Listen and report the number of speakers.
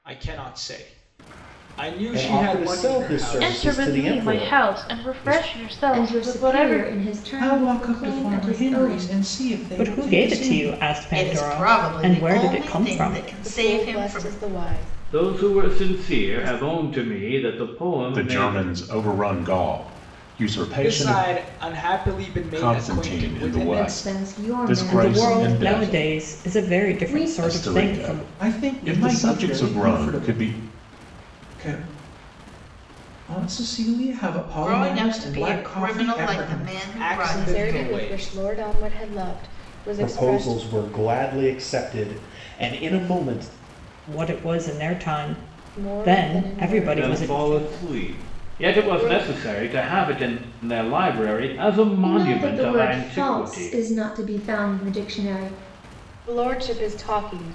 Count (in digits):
10